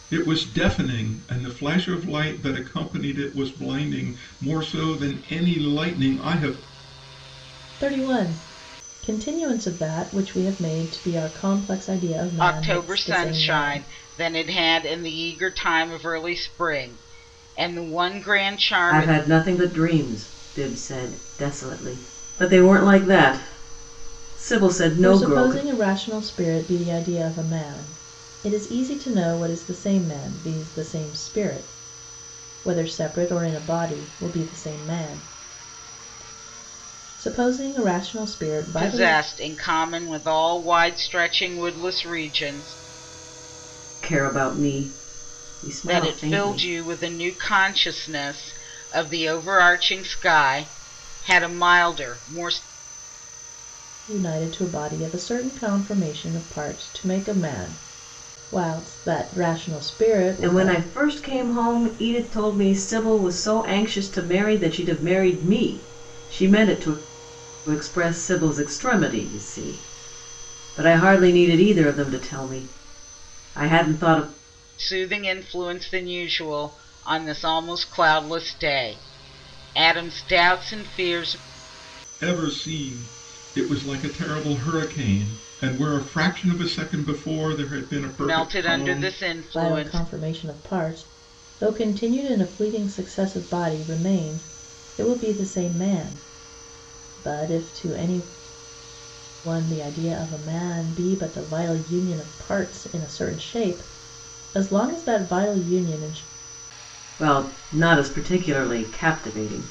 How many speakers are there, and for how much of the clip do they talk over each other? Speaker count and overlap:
4, about 5%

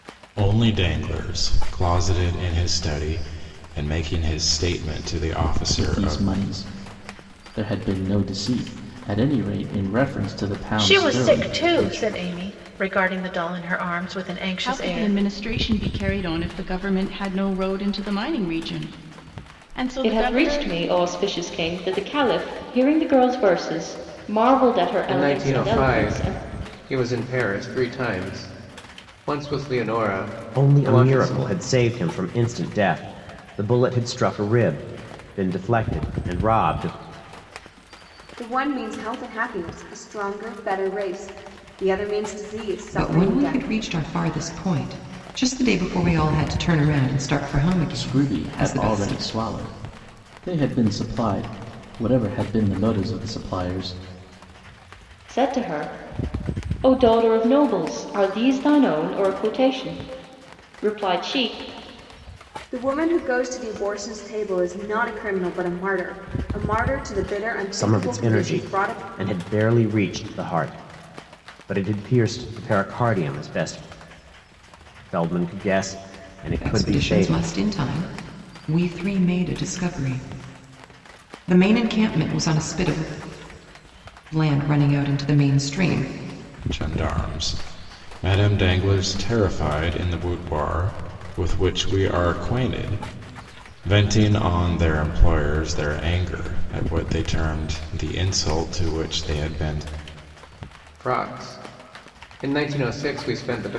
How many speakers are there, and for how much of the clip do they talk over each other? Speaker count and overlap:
9, about 10%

